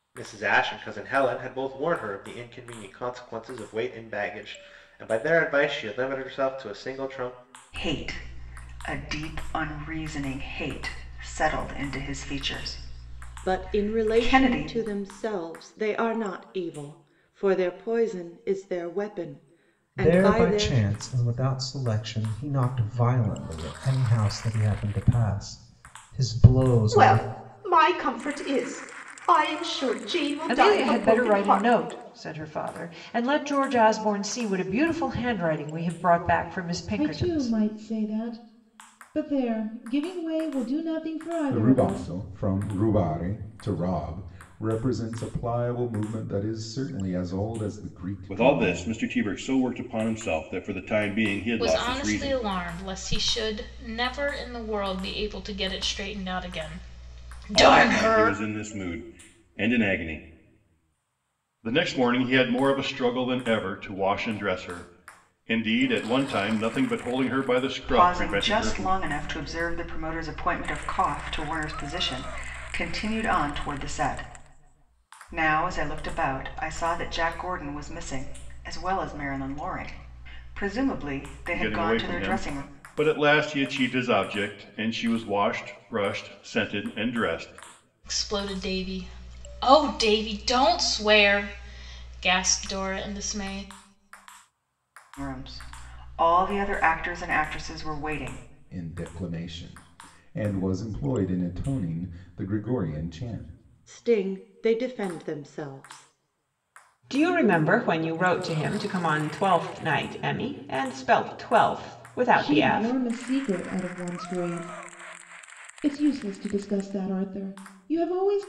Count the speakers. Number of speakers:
10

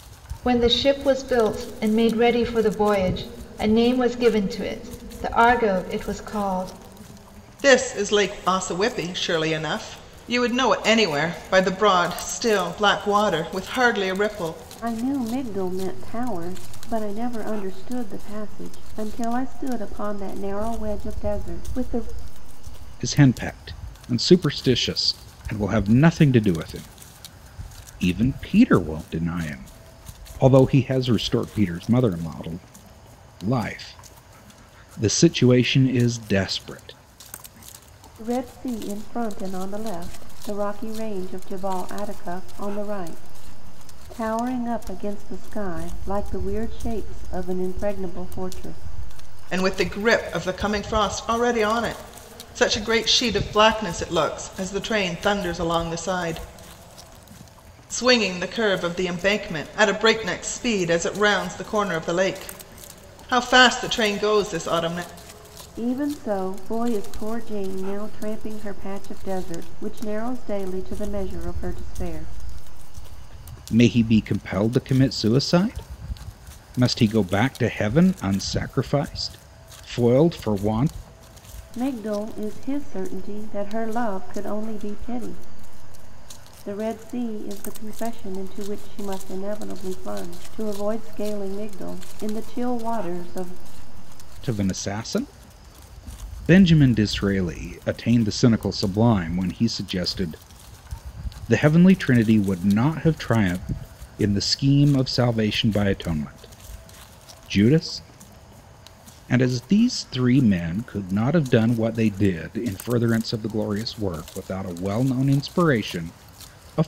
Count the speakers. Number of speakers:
4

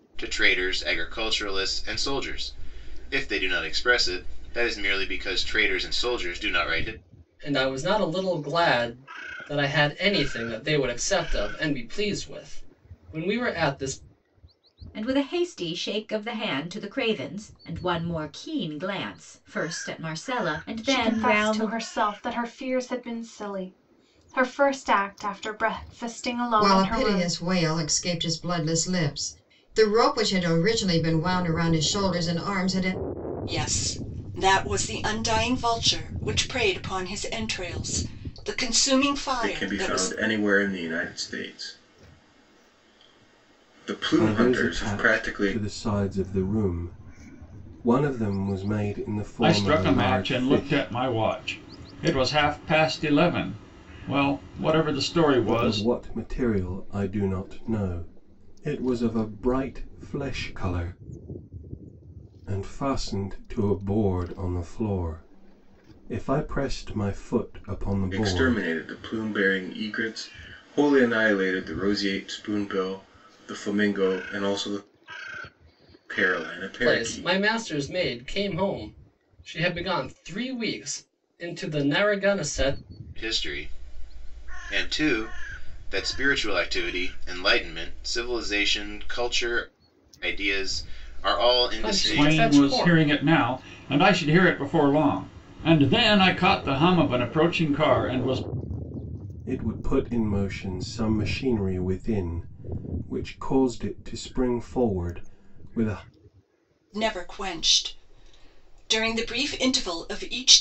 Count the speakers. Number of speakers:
9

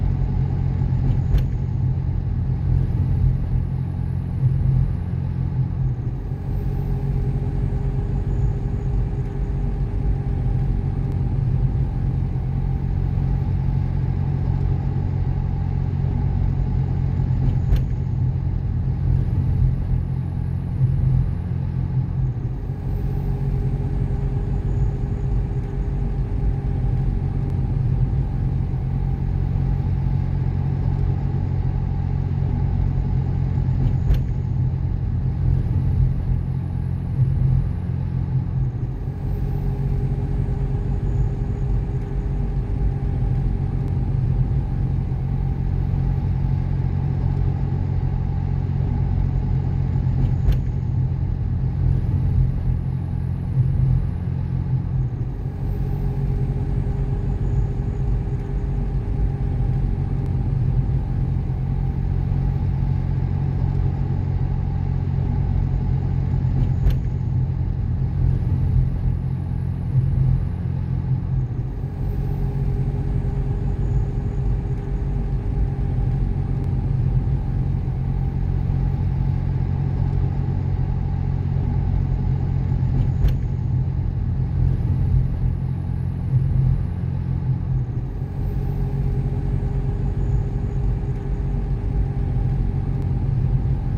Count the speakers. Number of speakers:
0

